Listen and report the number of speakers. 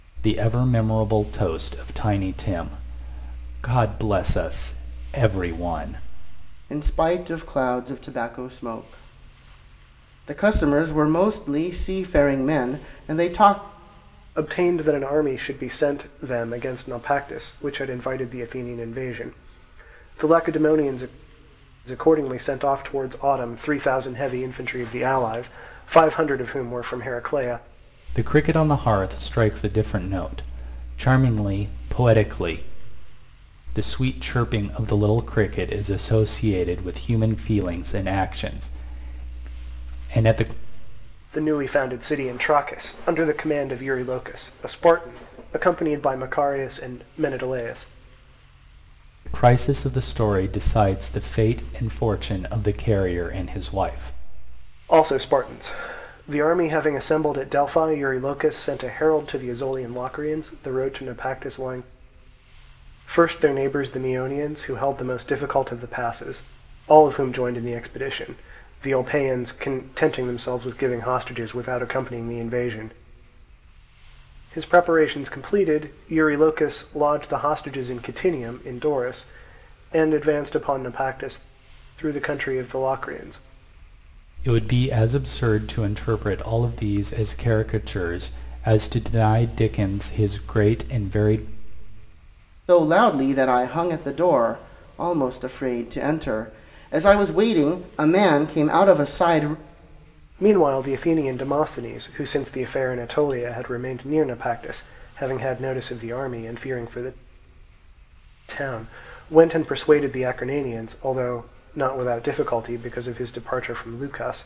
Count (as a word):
three